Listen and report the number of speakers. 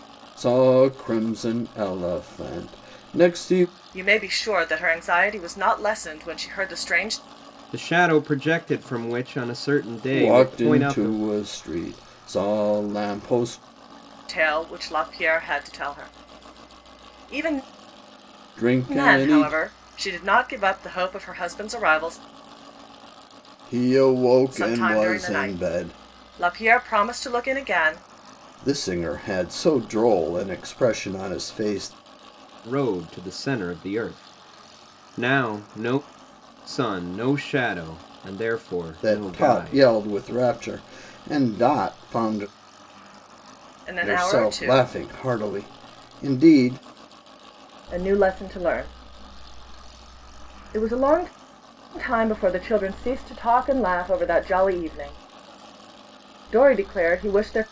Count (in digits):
3